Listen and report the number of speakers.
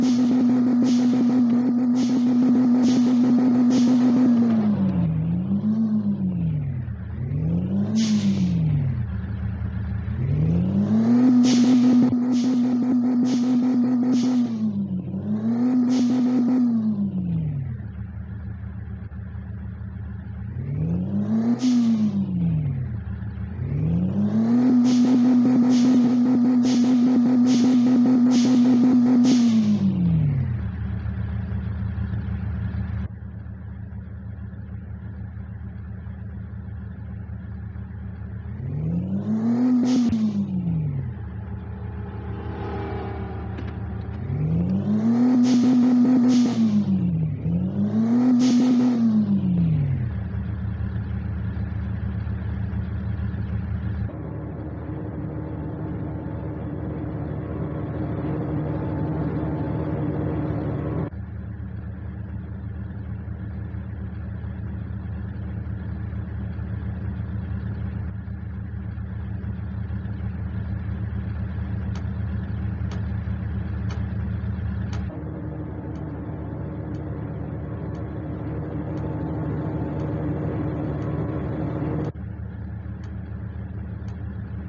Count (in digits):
0